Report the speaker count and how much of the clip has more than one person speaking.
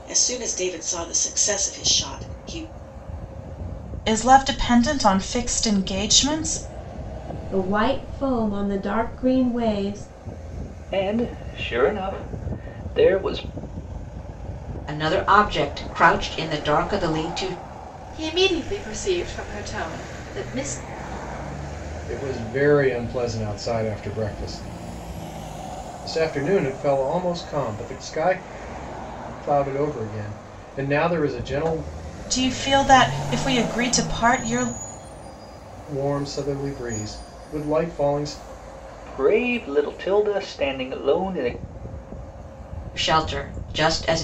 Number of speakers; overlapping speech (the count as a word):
seven, no overlap